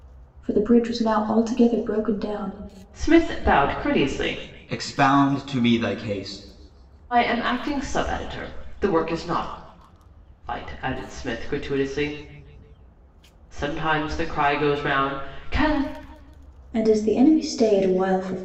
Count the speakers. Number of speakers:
3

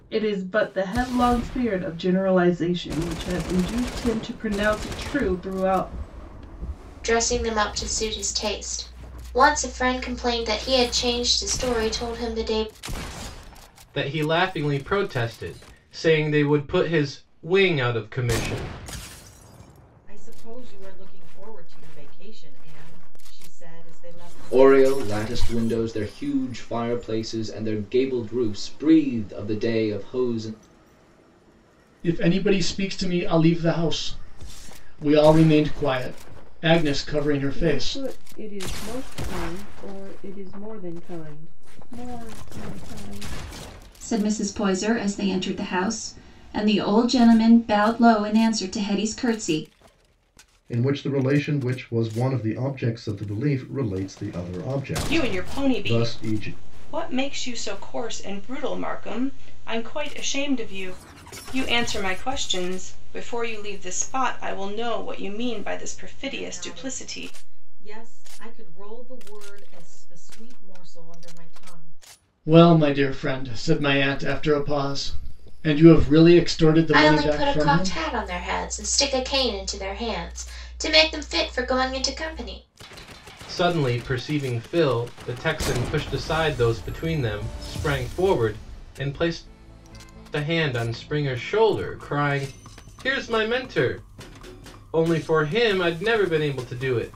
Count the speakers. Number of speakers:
10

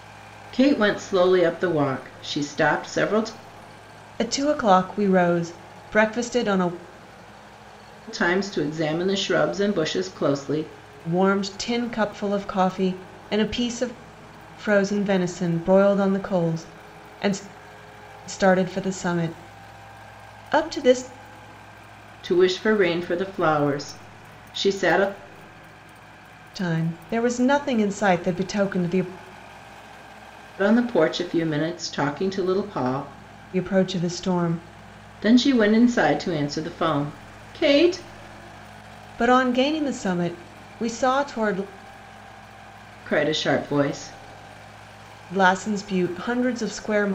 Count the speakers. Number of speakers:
2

